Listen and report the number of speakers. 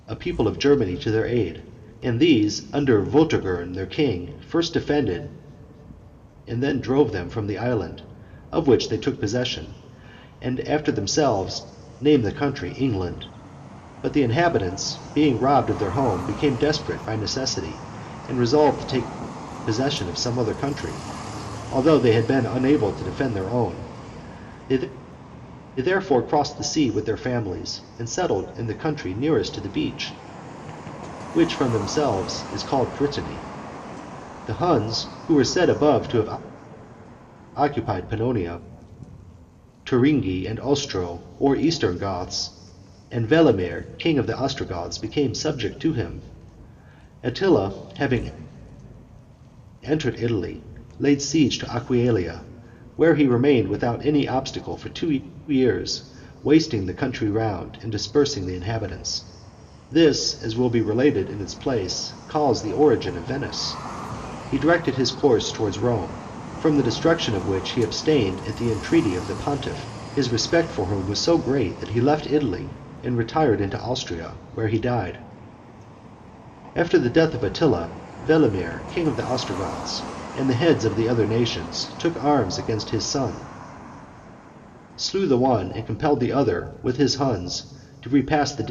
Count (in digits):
1